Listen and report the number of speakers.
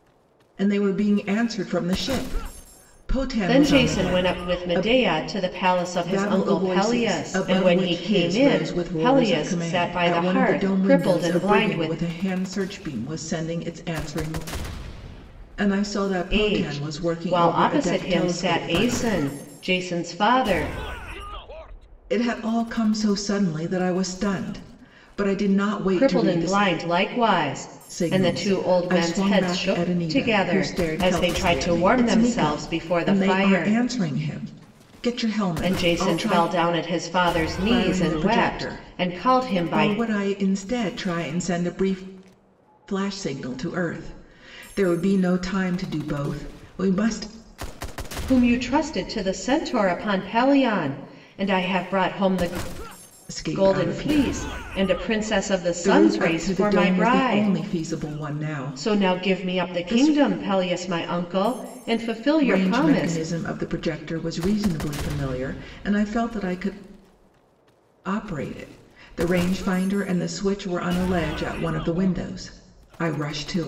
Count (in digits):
2